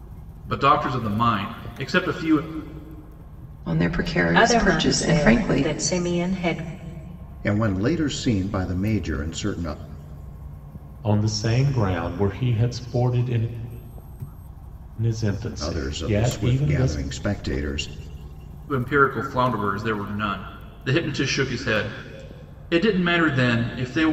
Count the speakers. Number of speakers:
five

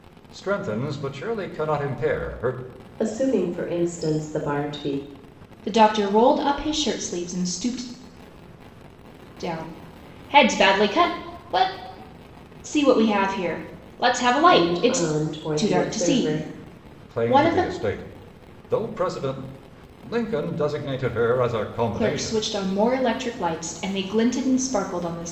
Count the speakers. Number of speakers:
three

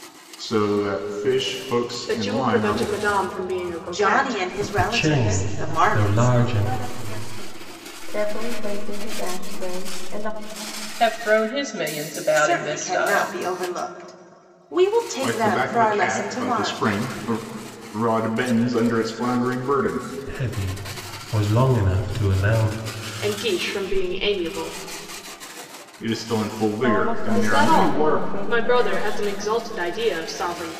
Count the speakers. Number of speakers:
seven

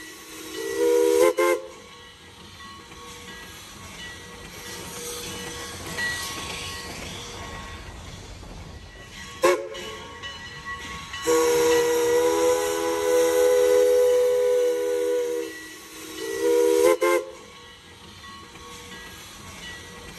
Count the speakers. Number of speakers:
zero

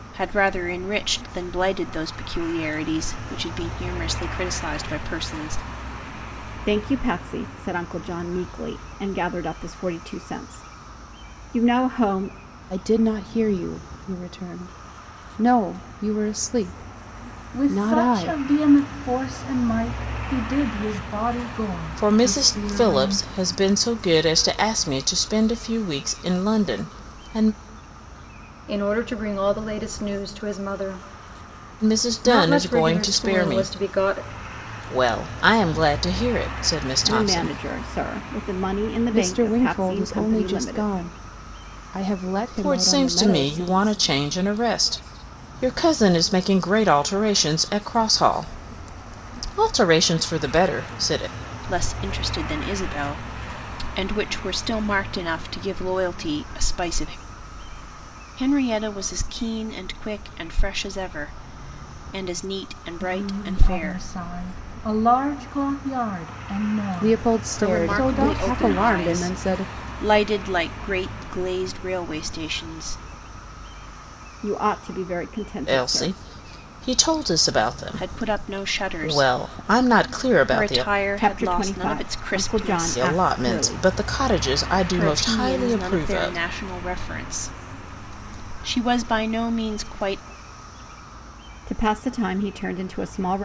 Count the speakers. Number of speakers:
six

